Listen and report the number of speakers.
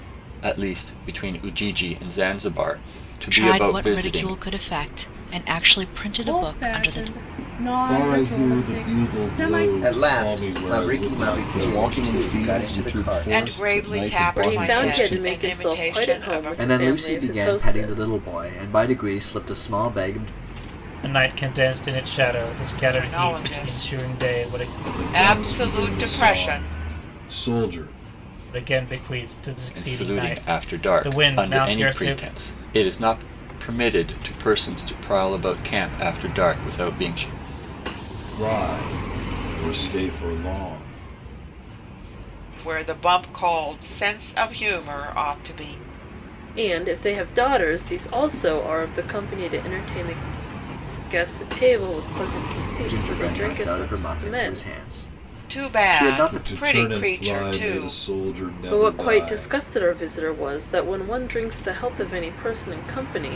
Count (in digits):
10